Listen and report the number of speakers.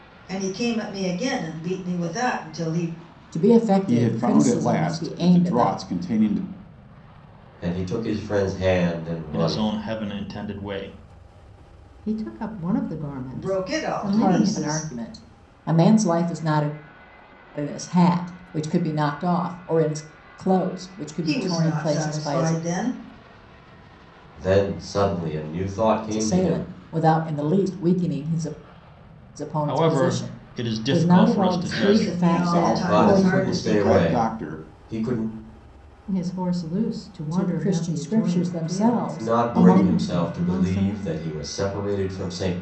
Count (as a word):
six